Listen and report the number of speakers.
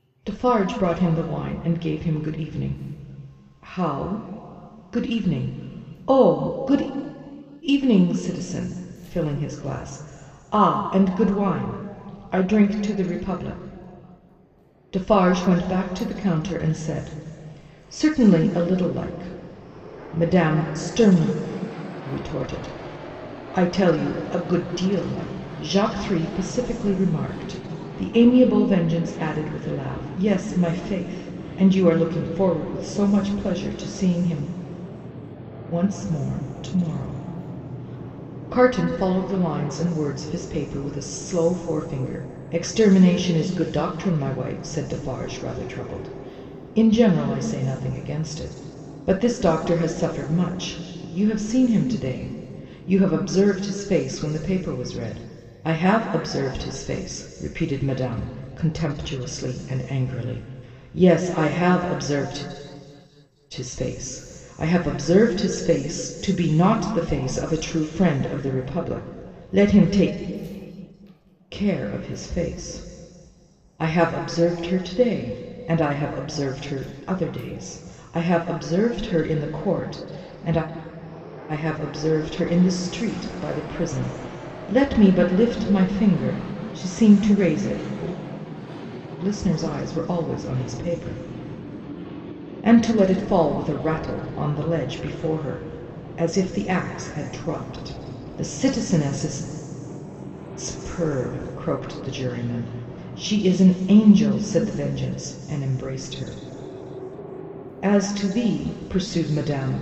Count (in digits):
1